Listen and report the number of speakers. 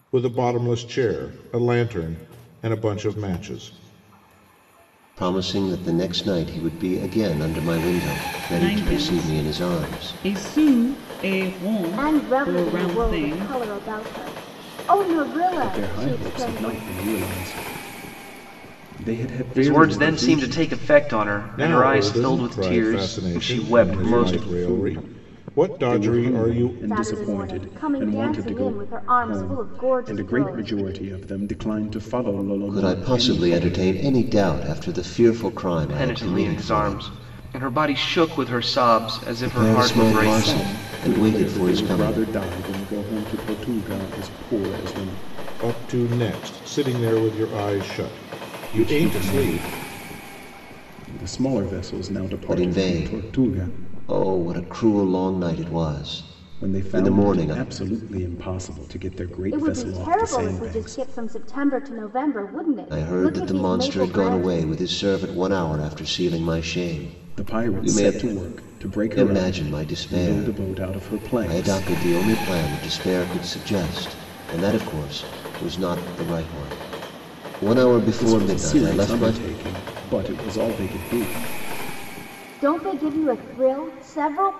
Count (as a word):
six